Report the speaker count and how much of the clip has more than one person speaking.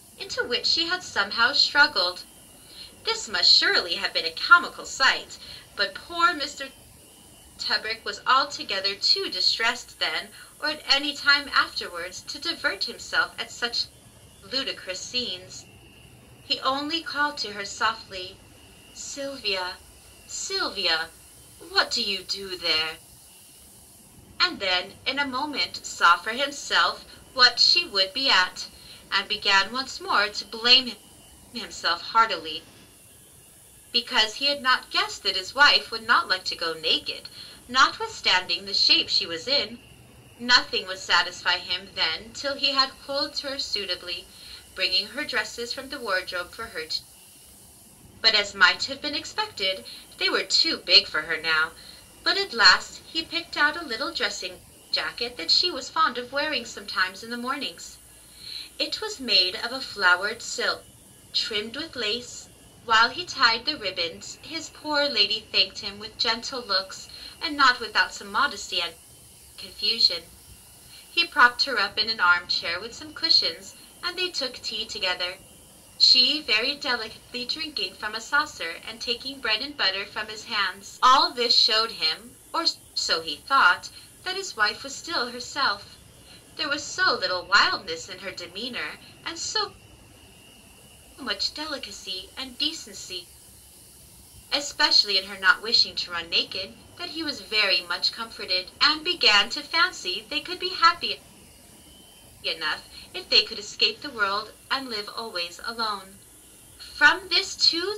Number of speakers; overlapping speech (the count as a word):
one, no overlap